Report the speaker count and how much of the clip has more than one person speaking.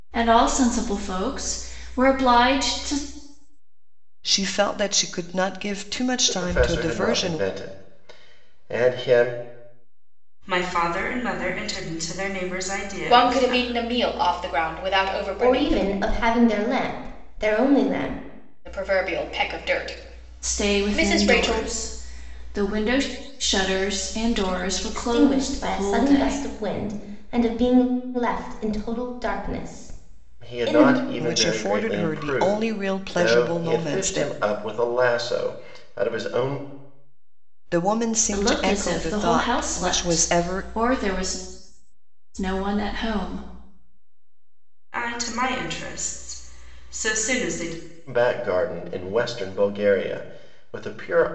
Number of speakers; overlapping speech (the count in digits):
6, about 22%